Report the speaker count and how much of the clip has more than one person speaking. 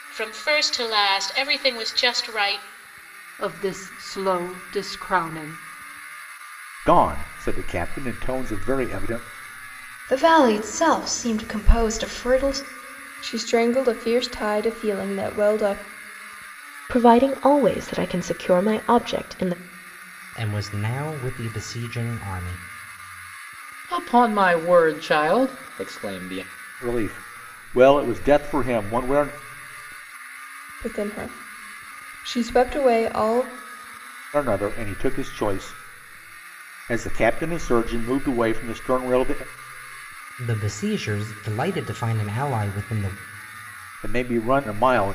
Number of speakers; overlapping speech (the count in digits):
8, no overlap